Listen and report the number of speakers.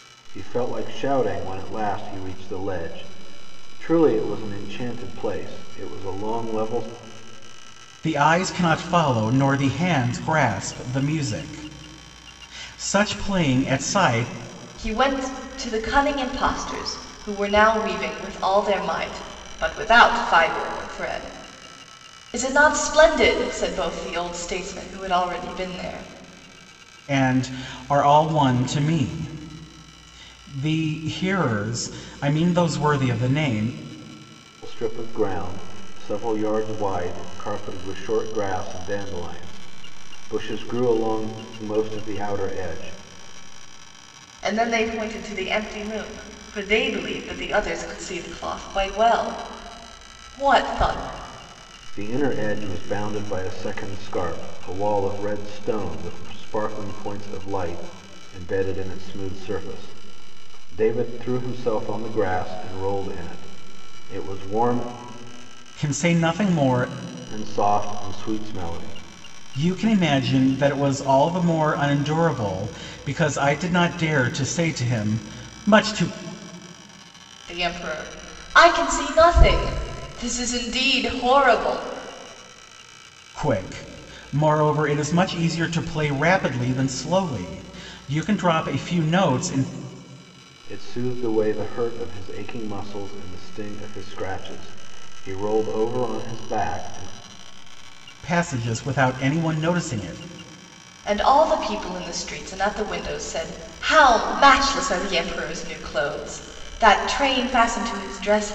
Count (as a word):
three